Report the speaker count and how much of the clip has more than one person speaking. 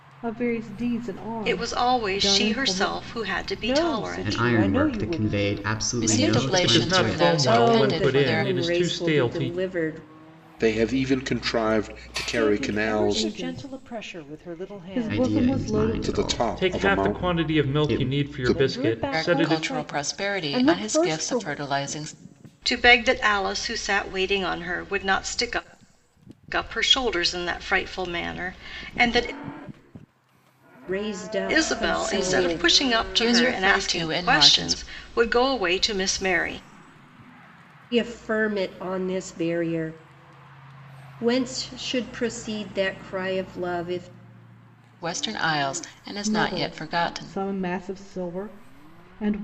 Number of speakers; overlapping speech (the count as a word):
eight, about 43%